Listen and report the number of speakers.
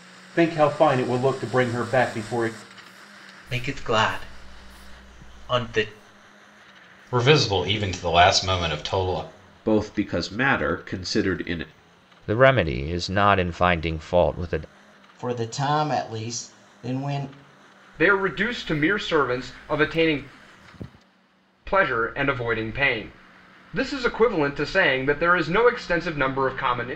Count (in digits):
7